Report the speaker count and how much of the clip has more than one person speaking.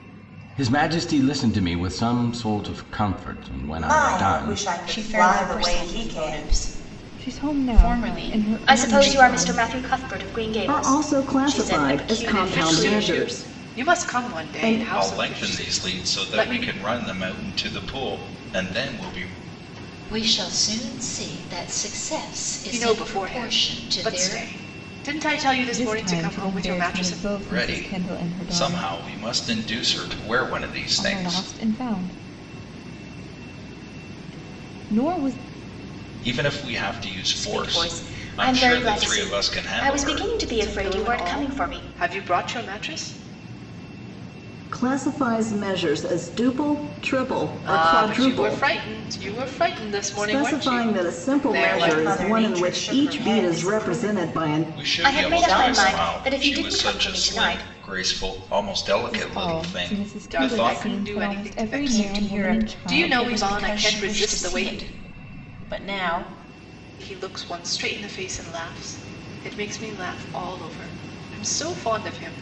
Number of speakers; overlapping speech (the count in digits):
9, about 48%